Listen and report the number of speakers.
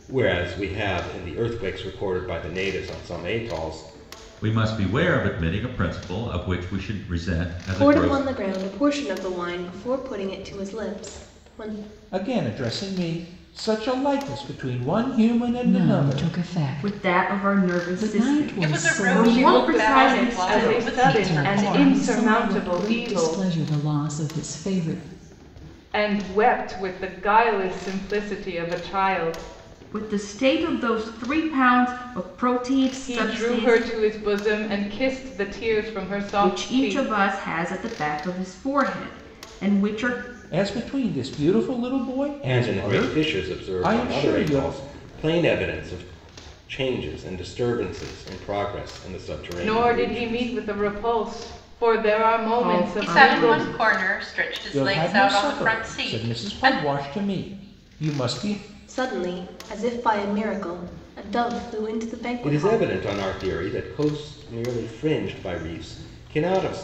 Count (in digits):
8